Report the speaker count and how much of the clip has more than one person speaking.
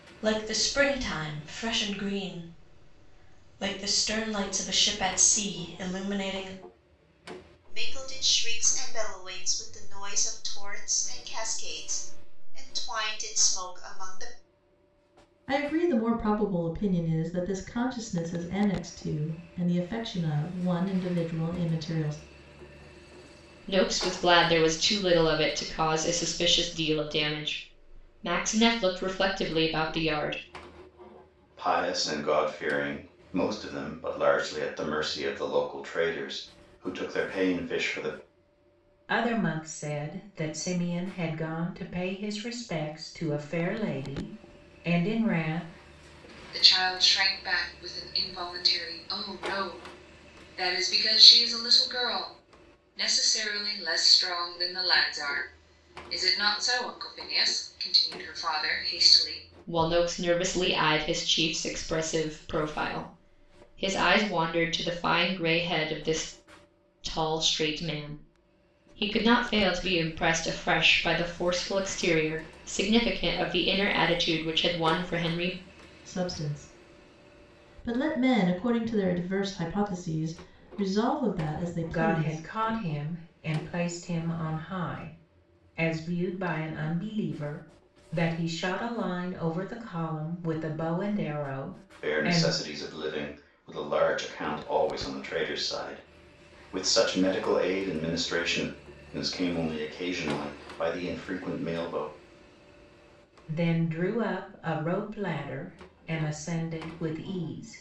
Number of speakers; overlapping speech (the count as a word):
seven, about 1%